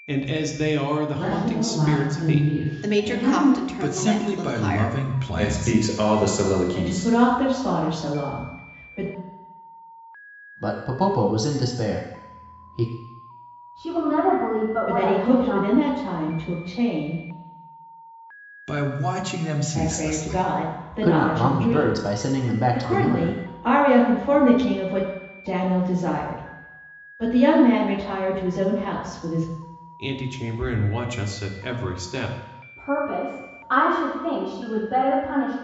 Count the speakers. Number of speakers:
8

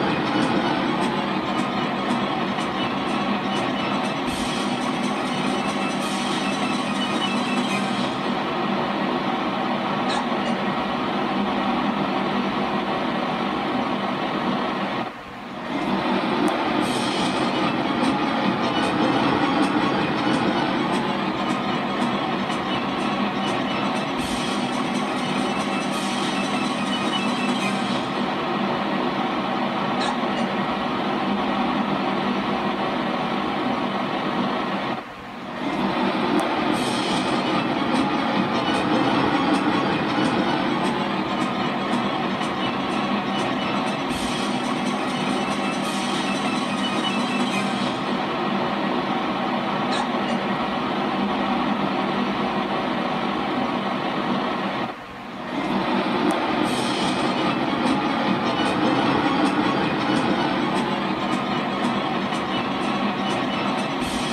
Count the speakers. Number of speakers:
0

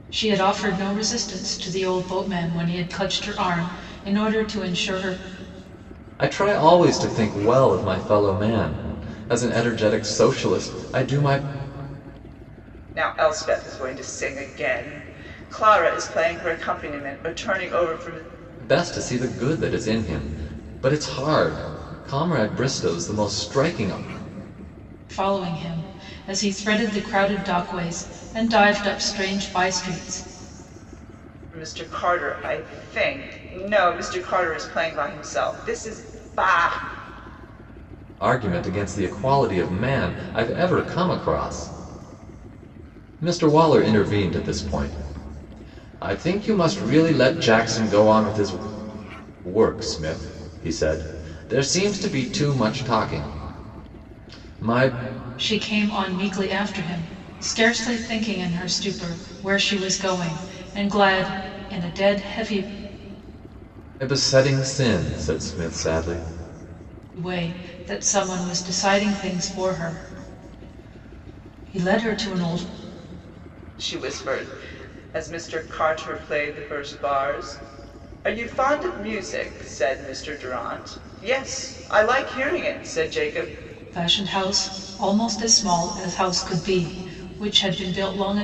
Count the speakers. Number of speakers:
3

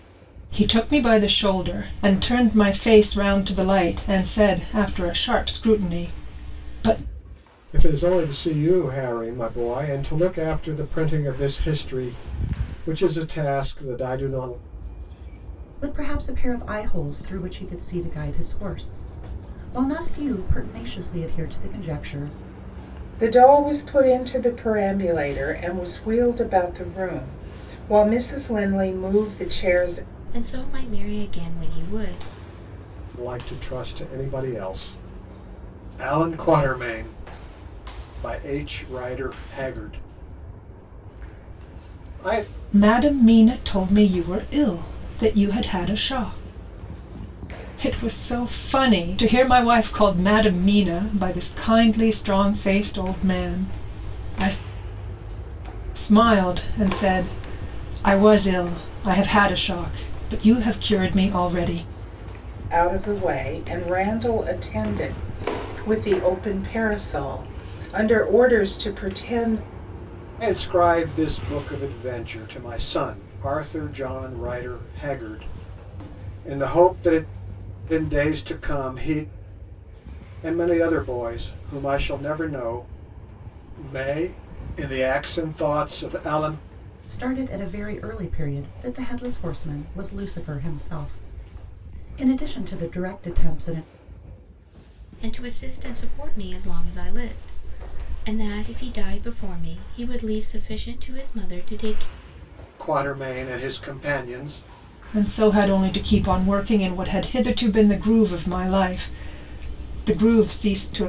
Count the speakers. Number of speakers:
5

